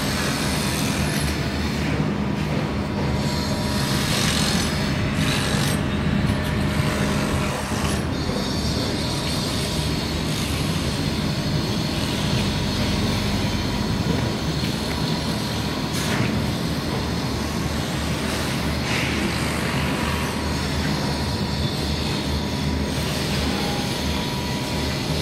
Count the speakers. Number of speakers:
zero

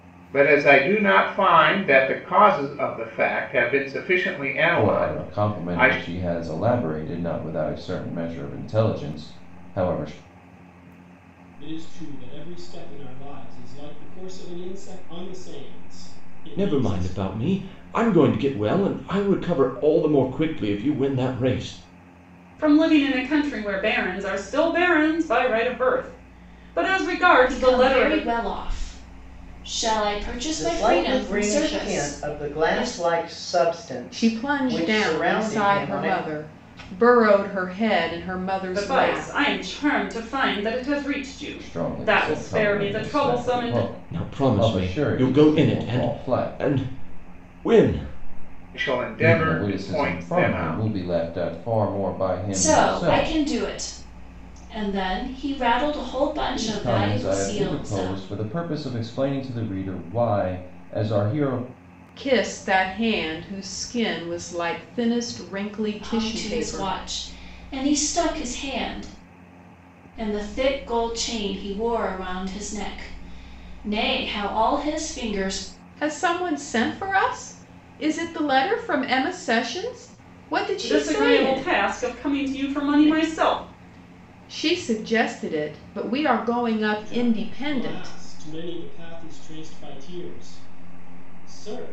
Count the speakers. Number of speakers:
eight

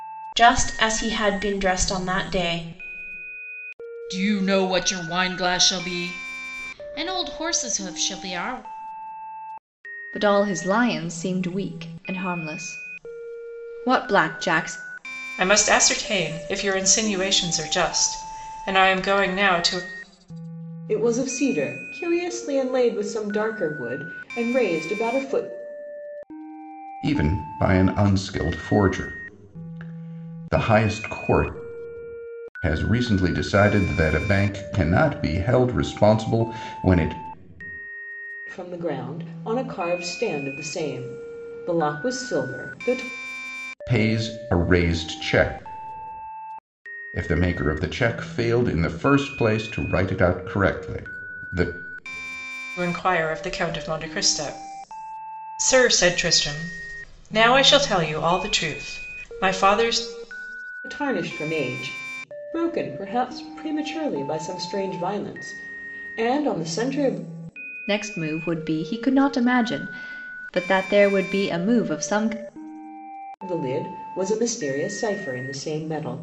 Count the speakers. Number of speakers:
six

